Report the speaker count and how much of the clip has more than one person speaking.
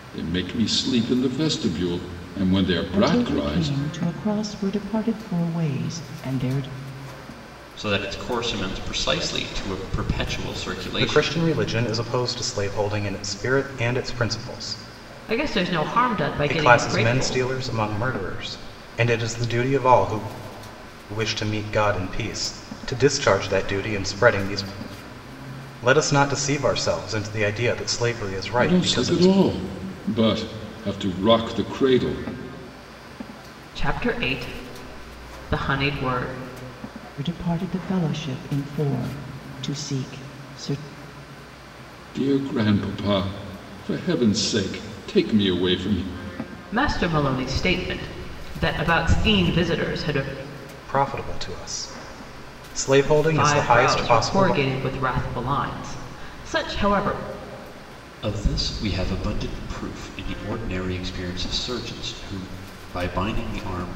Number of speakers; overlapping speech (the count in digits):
5, about 7%